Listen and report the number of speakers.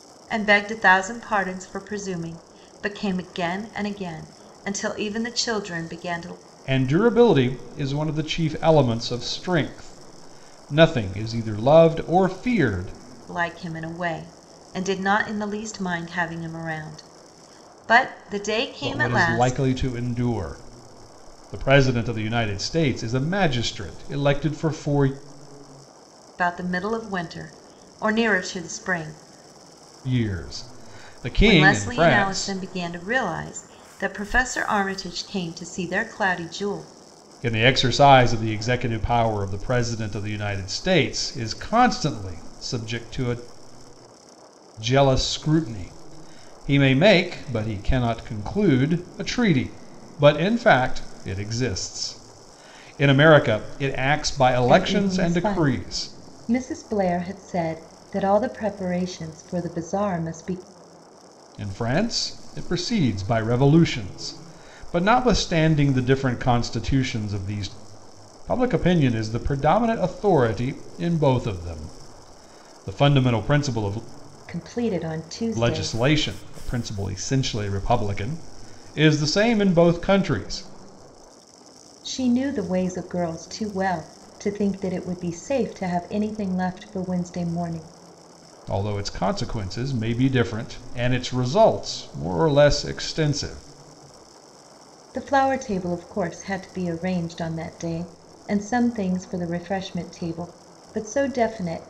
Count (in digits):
2